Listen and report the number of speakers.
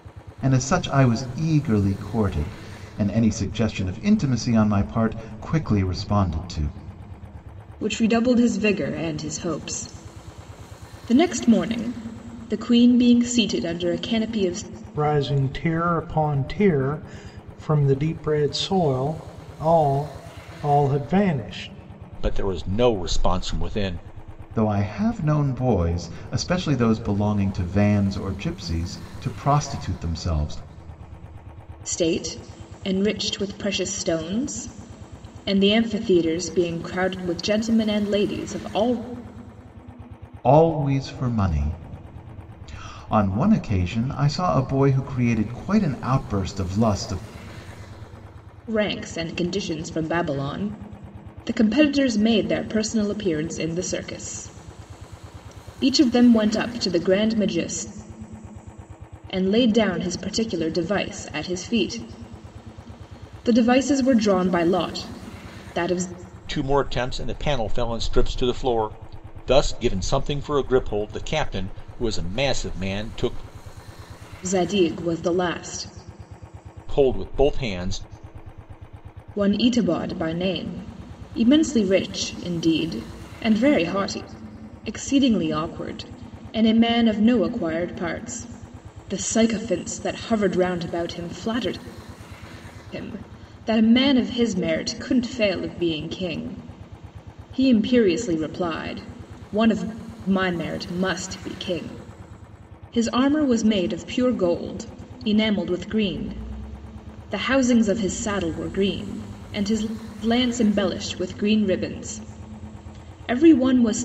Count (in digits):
4